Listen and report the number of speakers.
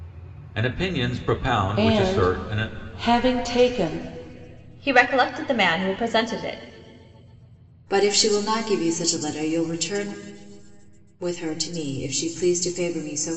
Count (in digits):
4